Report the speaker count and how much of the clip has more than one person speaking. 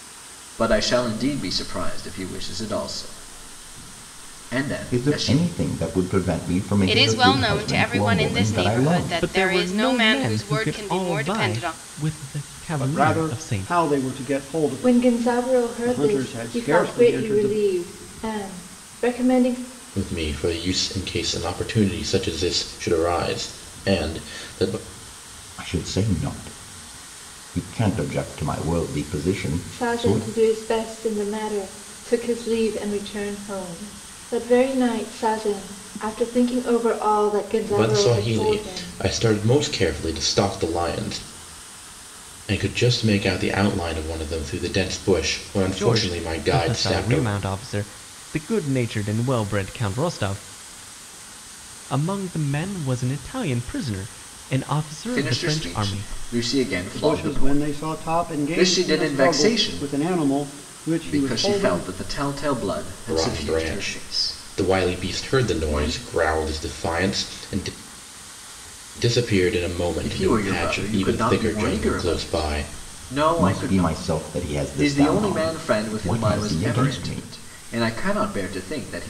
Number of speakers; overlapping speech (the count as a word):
seven, about 33%